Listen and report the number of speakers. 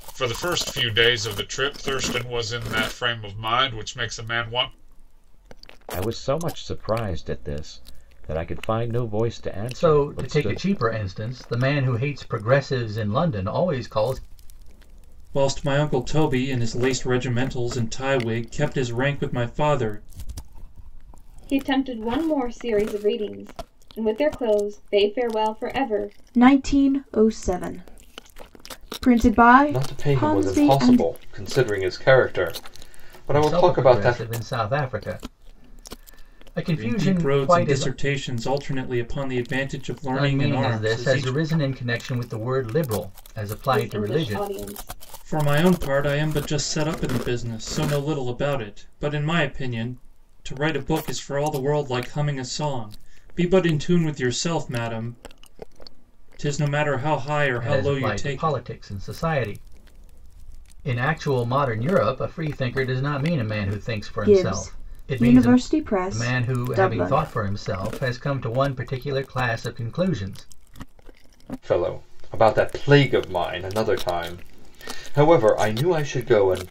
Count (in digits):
7